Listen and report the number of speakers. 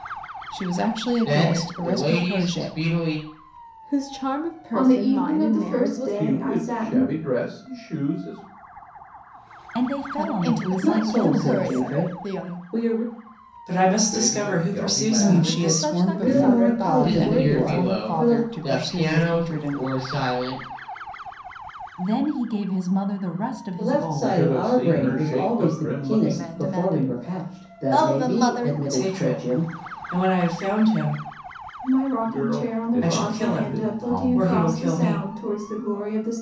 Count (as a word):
nine